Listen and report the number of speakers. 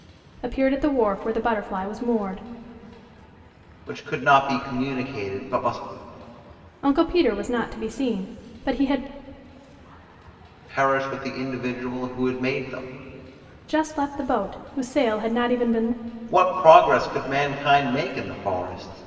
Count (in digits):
2